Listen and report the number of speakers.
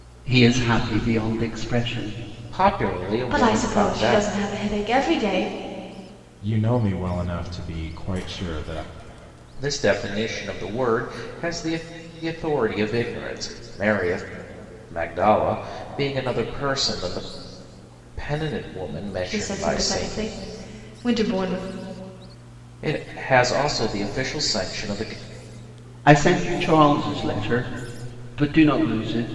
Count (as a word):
four